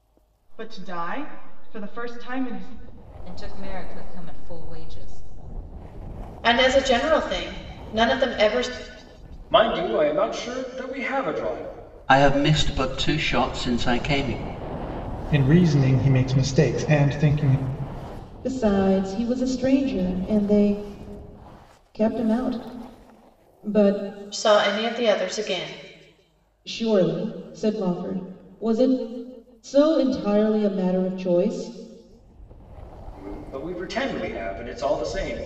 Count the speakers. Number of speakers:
seven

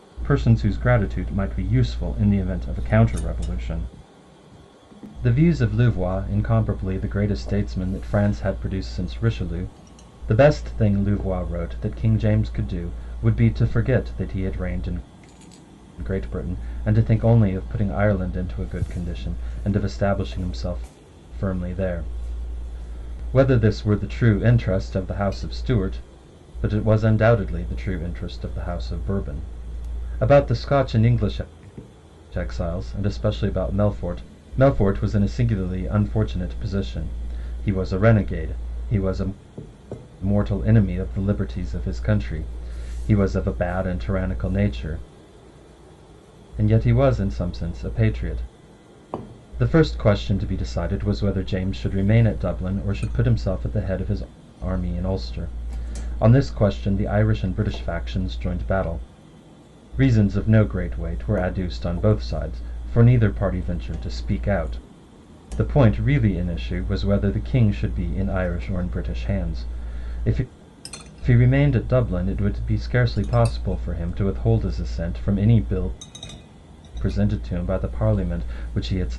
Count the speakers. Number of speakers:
one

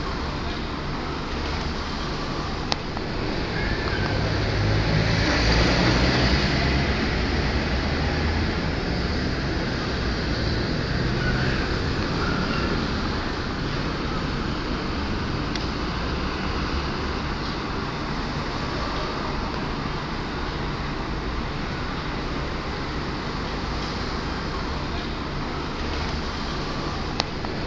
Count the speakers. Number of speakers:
zero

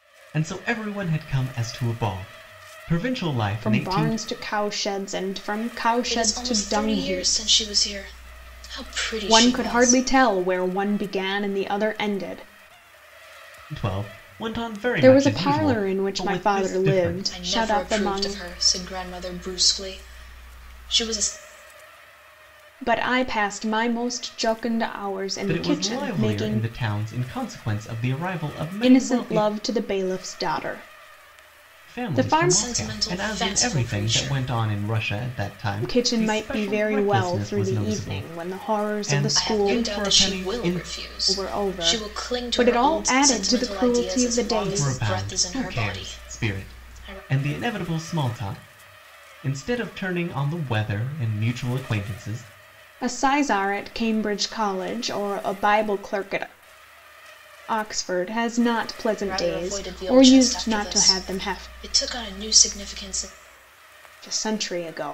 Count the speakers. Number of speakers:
three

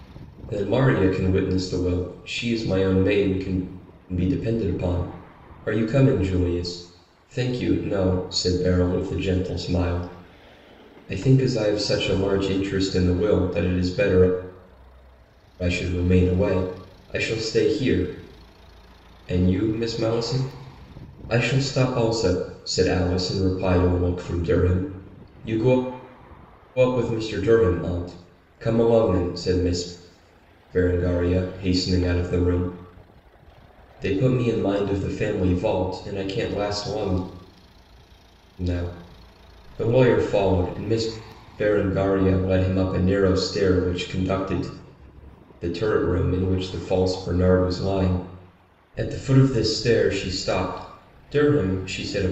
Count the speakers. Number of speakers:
one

